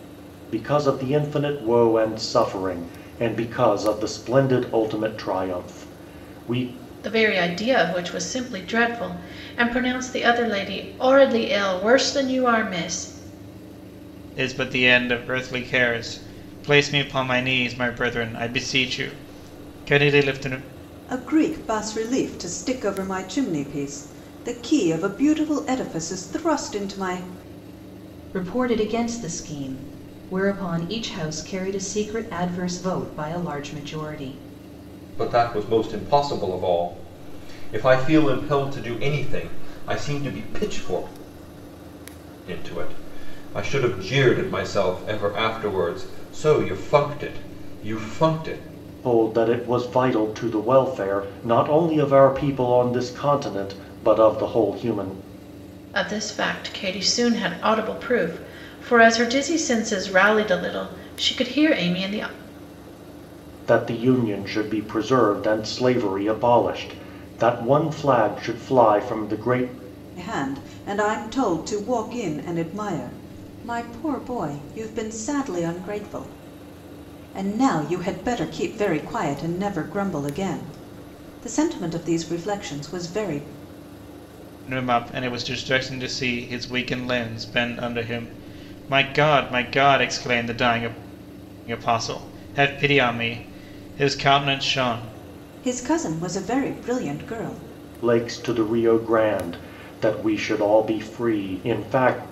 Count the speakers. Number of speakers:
6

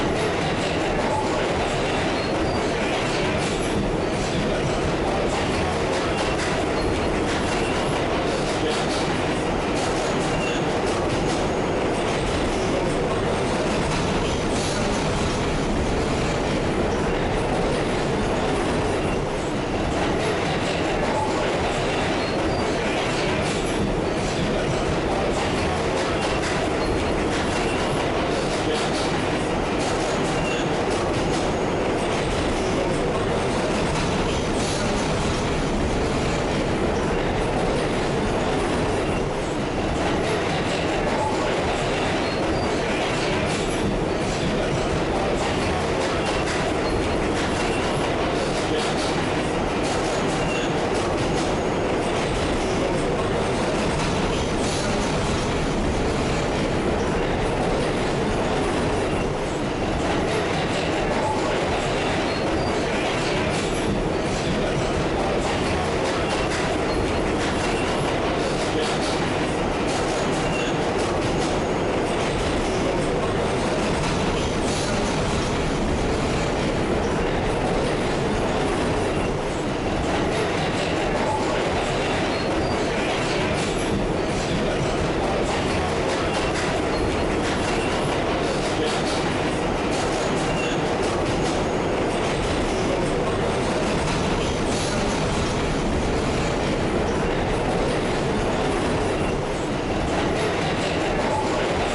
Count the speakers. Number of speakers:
0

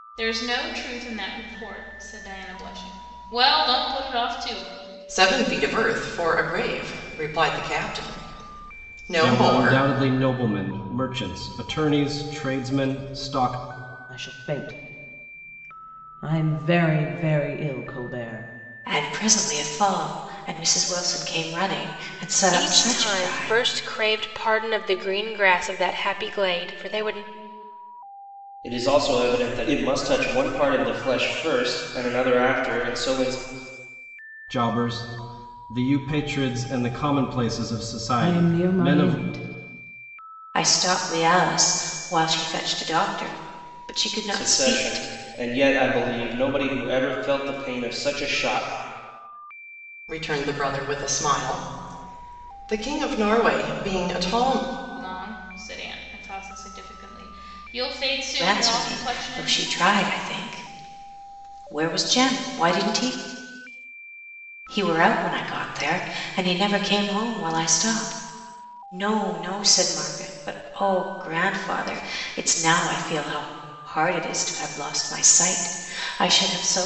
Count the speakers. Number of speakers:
7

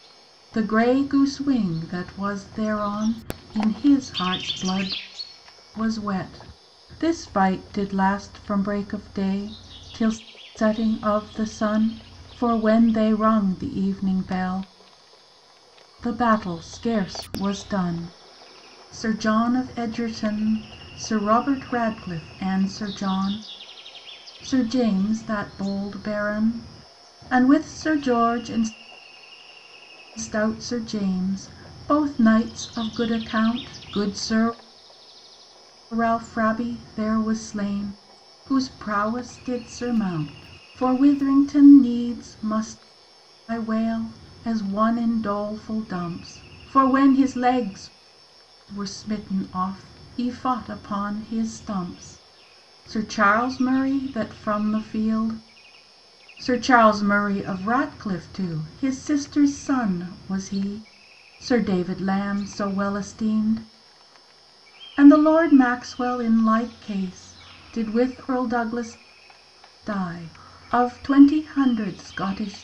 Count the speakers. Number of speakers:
1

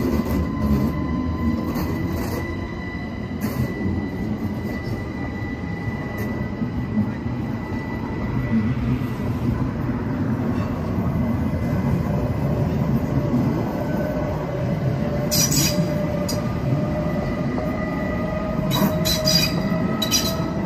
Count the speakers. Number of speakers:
0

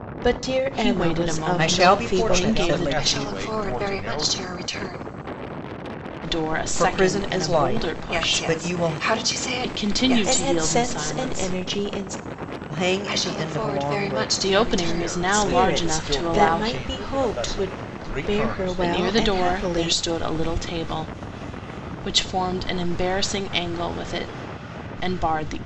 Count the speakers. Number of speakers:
5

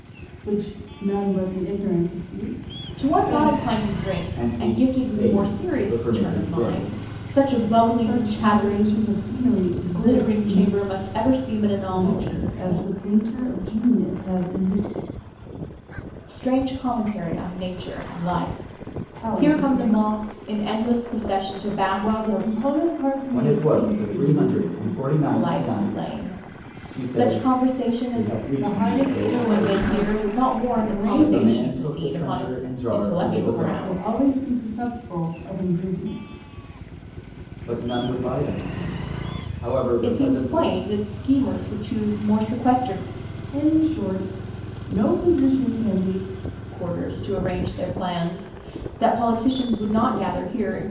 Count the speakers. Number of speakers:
3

